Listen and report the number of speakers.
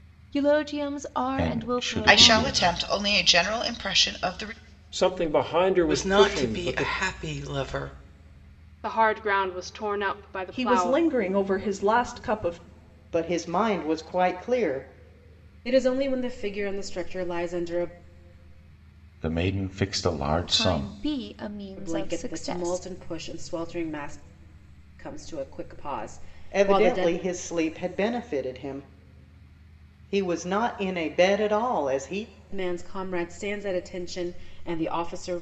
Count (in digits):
9